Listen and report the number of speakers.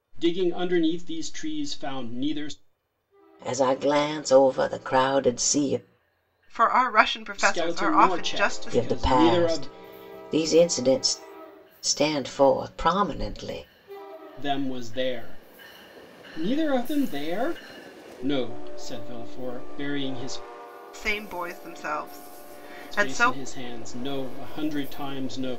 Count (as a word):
three